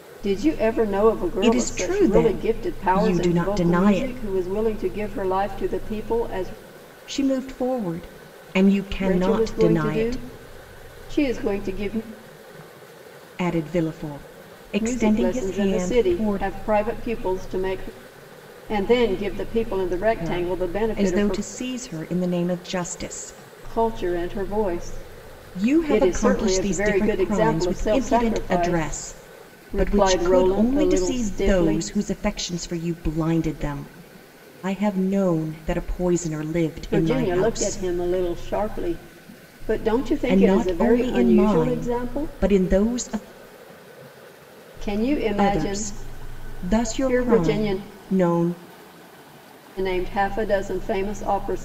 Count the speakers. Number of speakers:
2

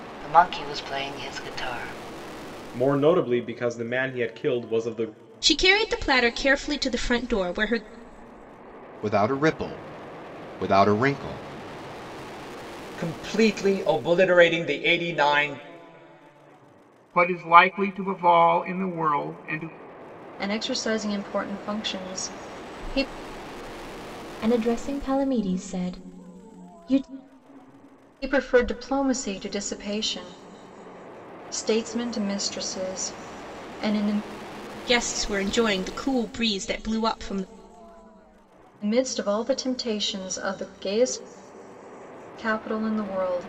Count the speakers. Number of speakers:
8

